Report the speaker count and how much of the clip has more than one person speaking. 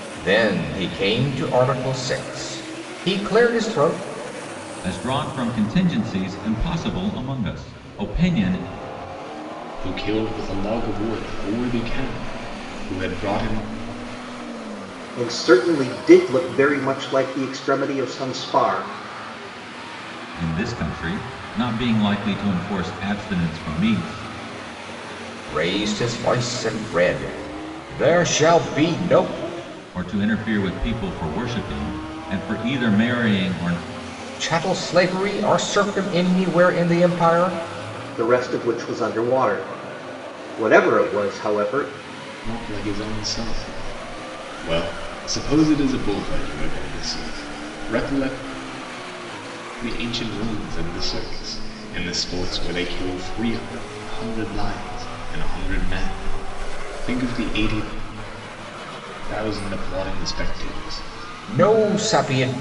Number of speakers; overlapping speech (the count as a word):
four, no overlap